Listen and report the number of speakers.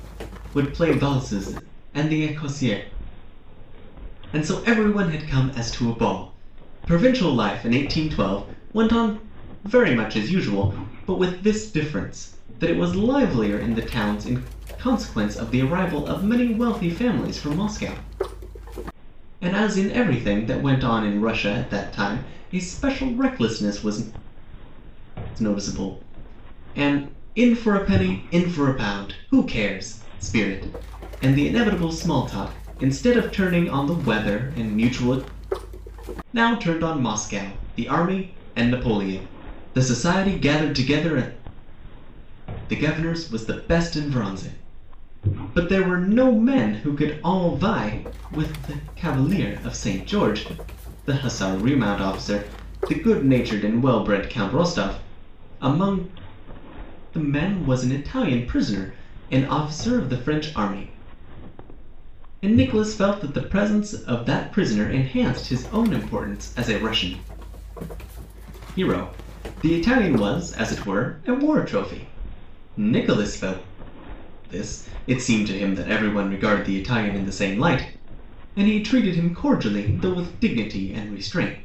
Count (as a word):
one